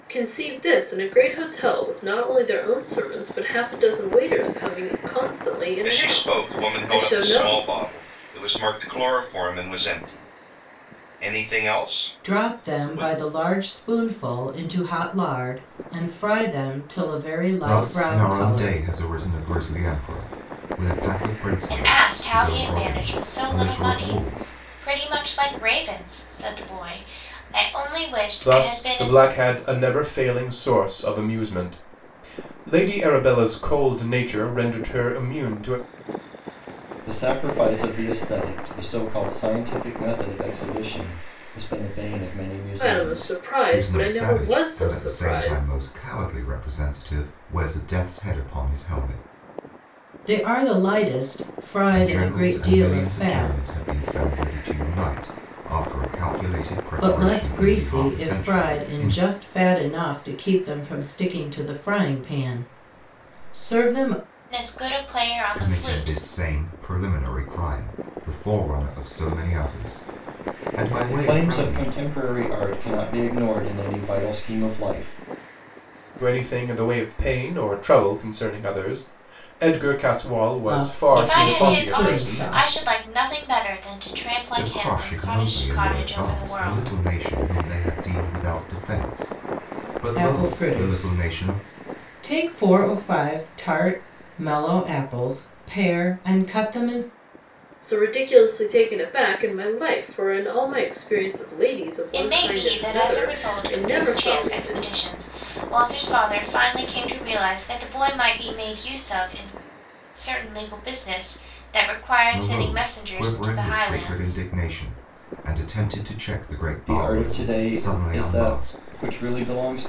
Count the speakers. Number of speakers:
7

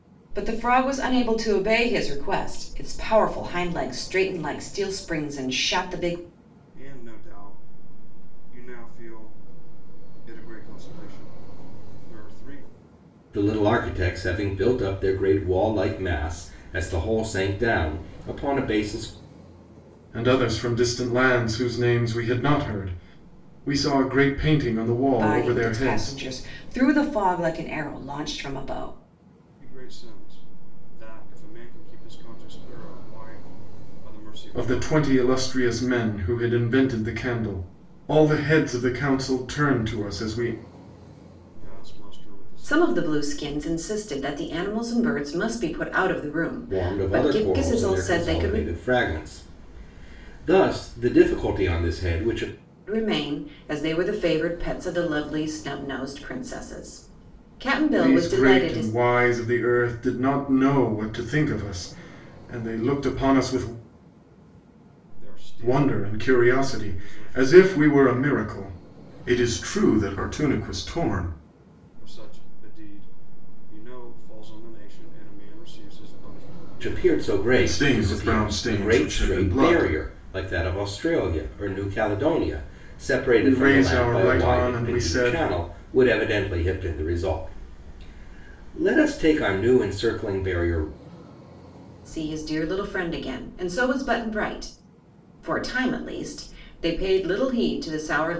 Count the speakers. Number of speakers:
4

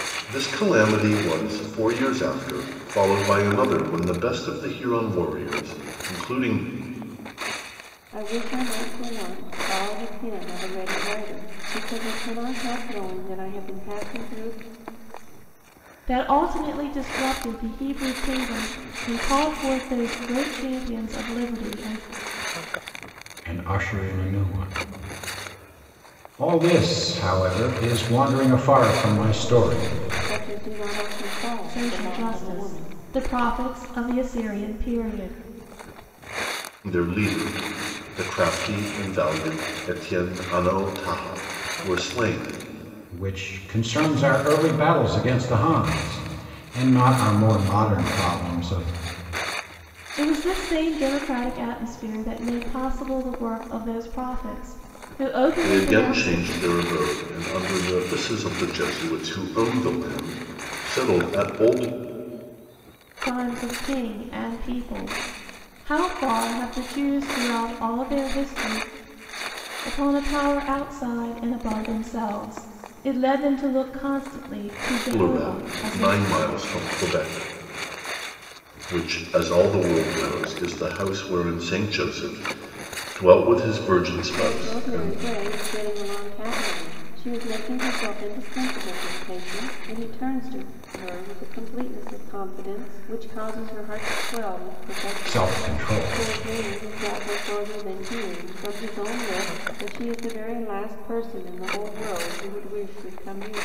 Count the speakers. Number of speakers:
4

